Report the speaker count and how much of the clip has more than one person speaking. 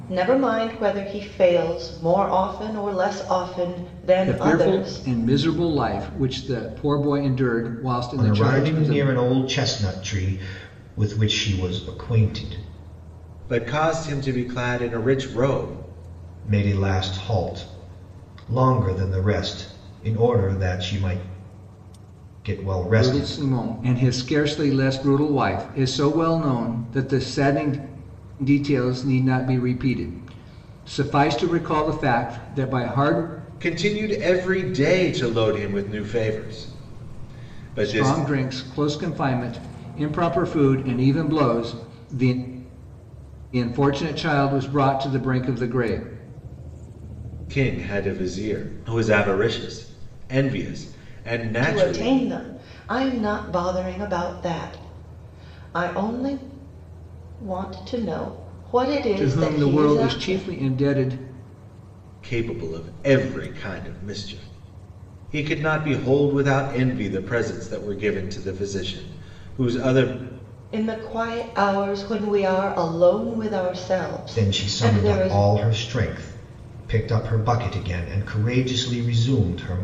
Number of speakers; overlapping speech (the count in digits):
4, about 7%